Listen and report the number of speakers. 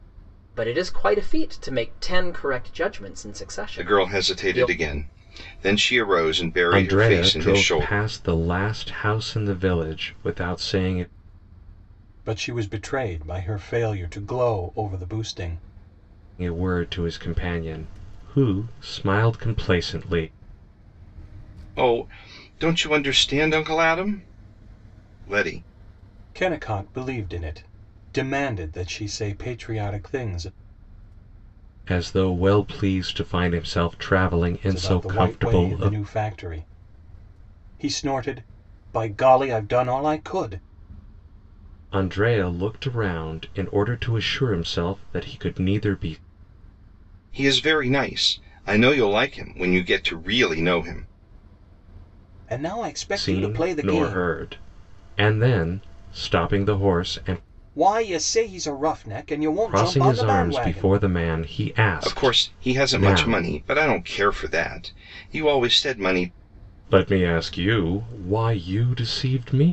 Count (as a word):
four